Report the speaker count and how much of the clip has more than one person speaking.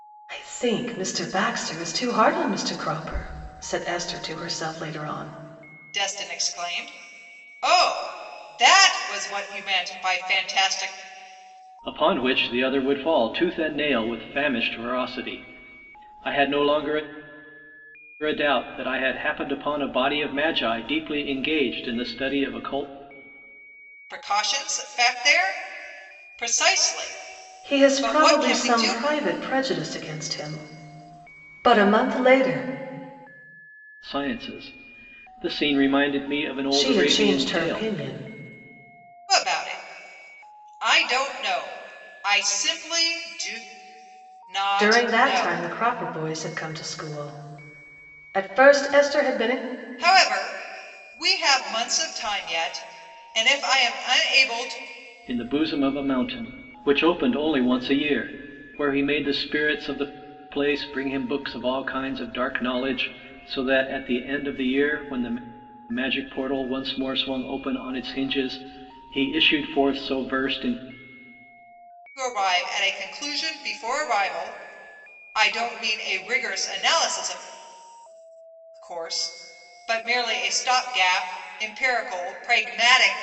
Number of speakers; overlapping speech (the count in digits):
3, about 4%